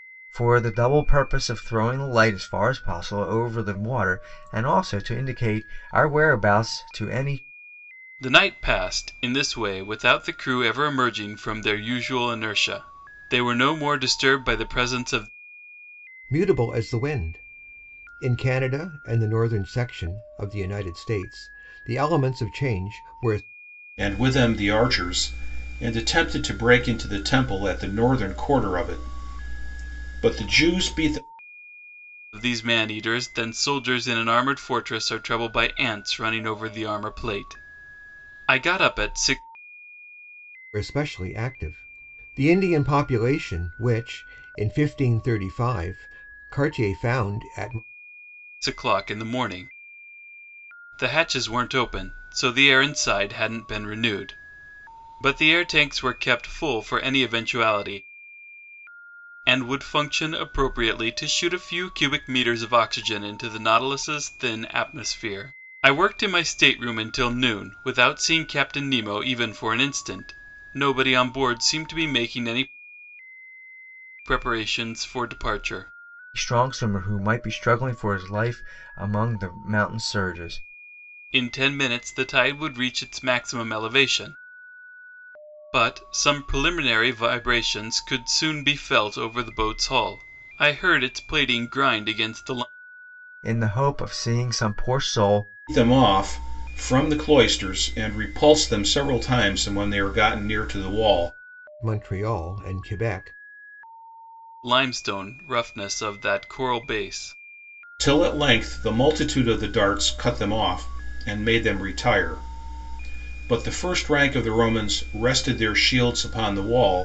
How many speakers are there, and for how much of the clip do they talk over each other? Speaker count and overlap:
4, no overlap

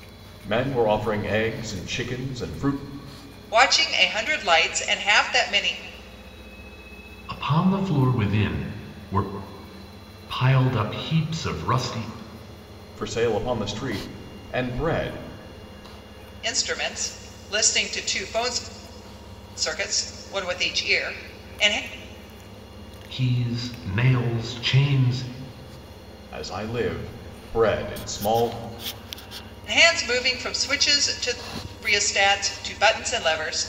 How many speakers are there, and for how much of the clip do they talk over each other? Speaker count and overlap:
3, no overlap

